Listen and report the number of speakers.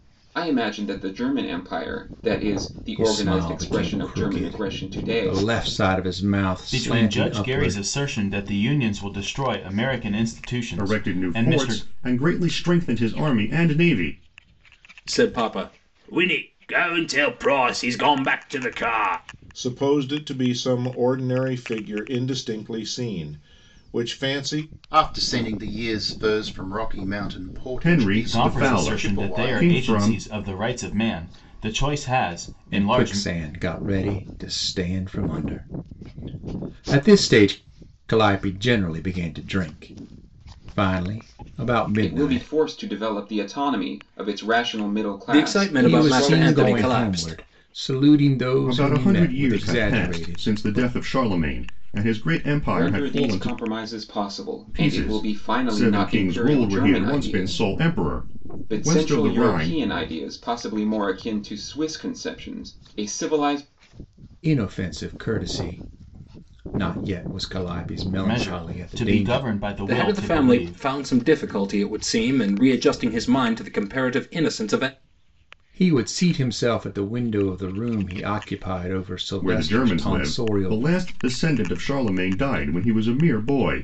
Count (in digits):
7